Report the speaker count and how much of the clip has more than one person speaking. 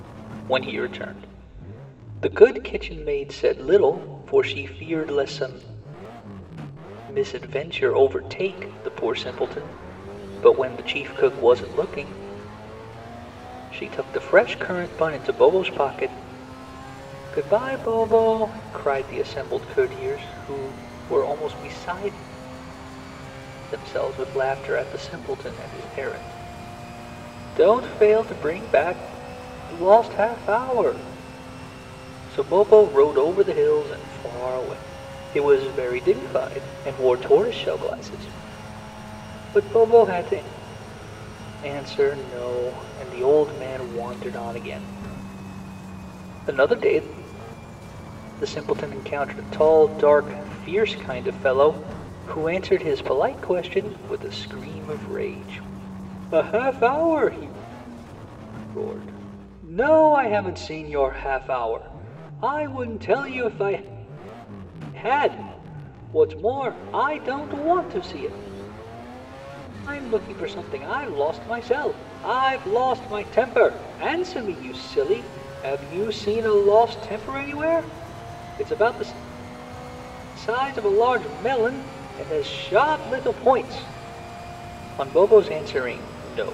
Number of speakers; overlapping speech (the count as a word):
one, no overlap